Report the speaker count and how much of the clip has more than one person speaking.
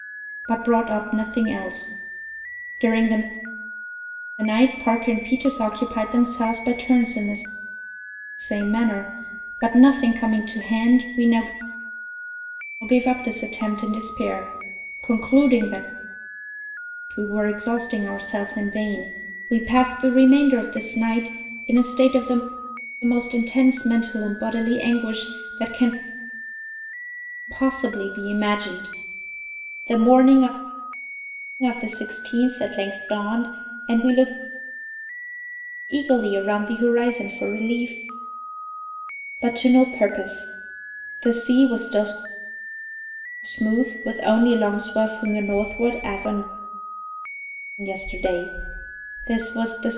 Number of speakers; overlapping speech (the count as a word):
one, no overlap